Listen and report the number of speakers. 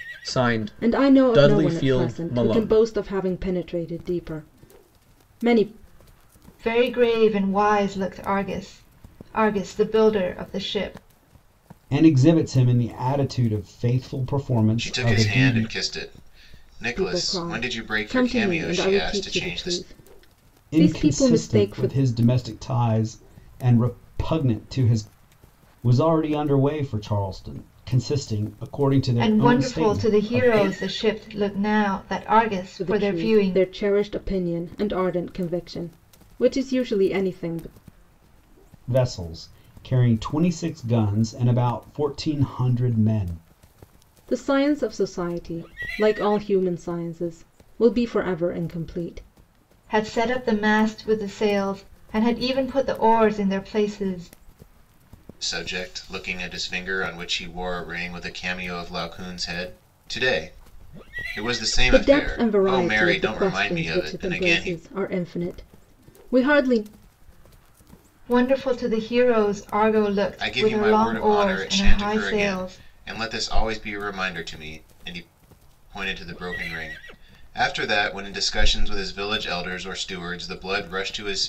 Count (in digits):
5